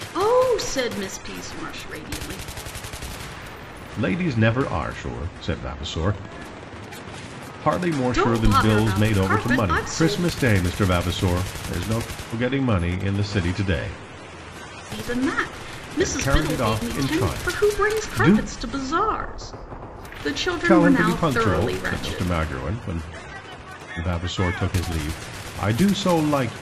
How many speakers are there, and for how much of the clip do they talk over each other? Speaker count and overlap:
2, about 24%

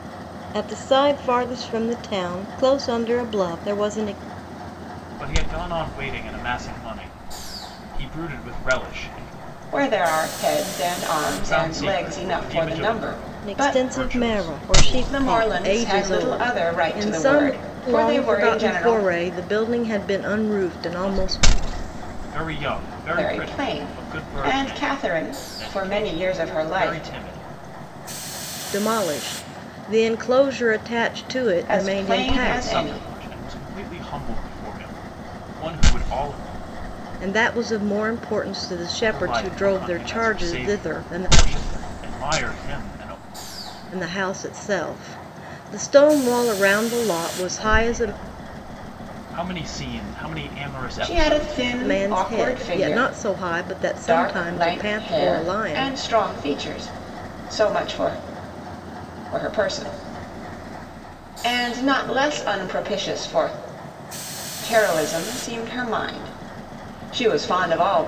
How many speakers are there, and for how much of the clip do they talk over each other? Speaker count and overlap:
3, about 29%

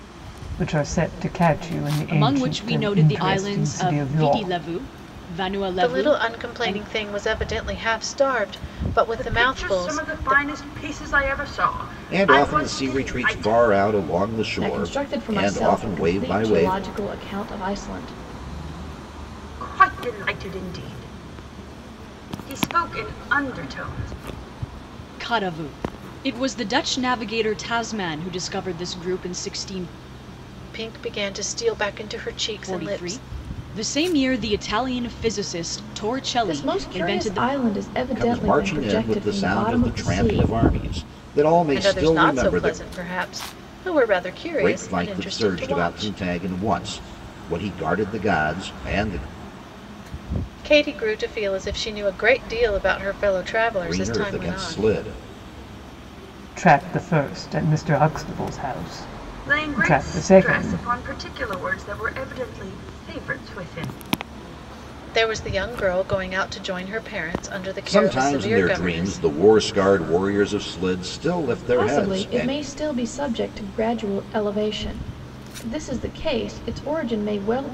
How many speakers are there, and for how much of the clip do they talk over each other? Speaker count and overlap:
6, about 27%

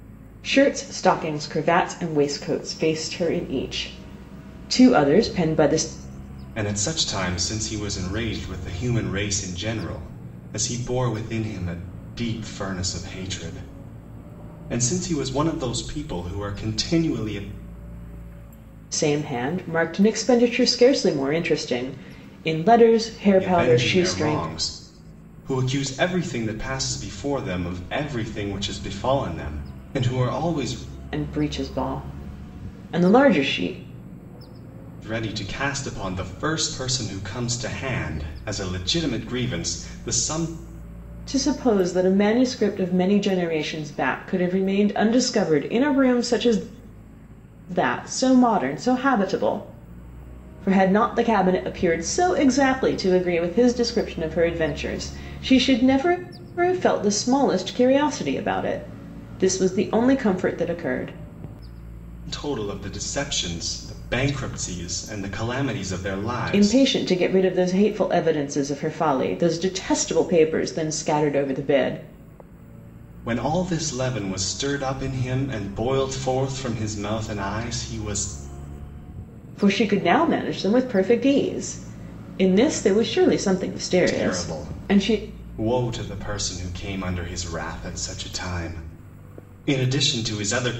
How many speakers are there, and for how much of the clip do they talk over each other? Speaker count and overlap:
2, about 3%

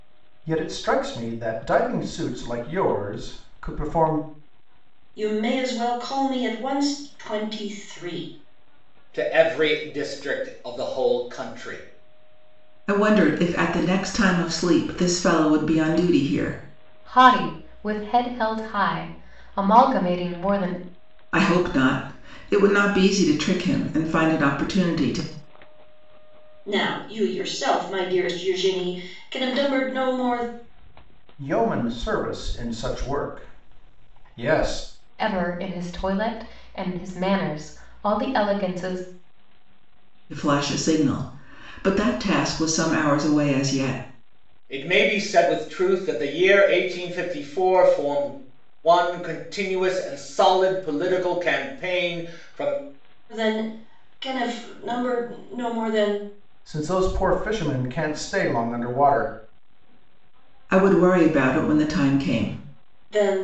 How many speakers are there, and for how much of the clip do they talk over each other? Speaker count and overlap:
5, no overlap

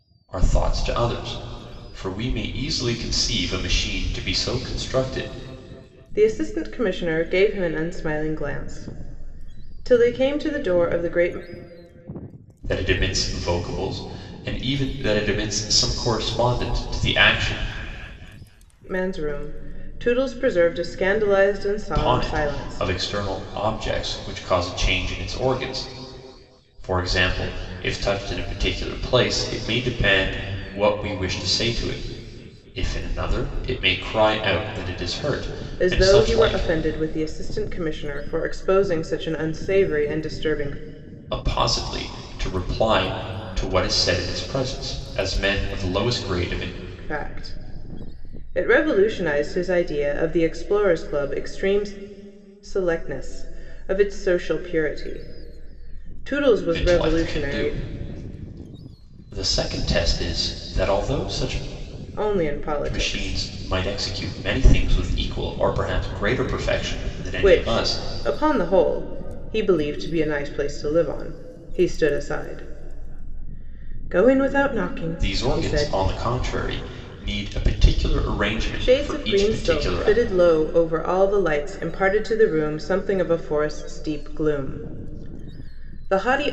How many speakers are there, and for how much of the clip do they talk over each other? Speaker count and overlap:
2, about 7%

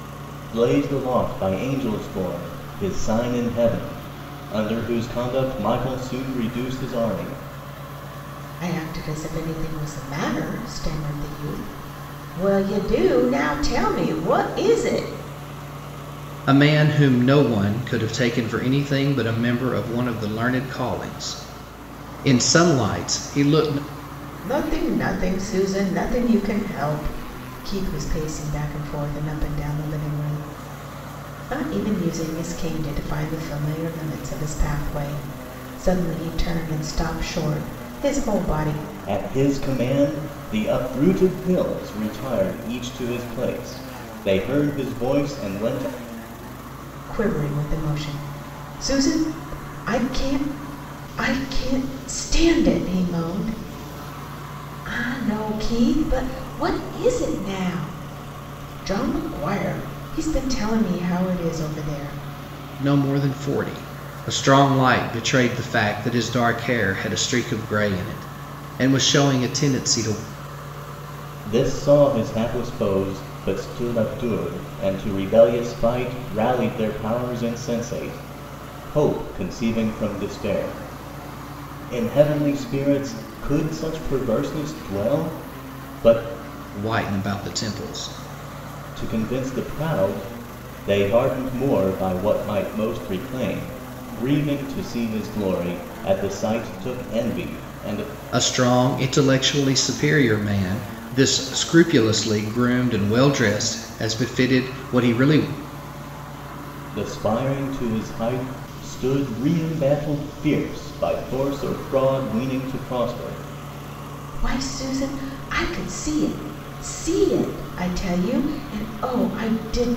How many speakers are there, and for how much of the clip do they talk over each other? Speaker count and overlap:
3, no overlap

